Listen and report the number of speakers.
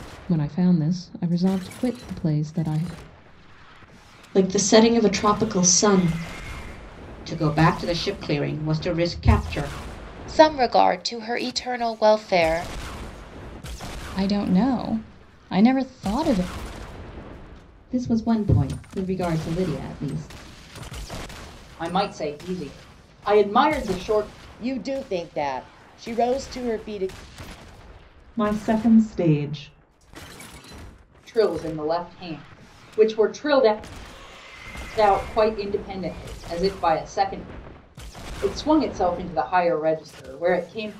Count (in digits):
9